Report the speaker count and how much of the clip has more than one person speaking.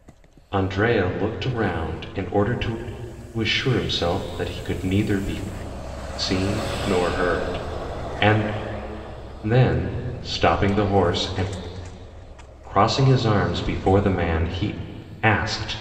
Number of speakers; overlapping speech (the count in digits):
1, no overlap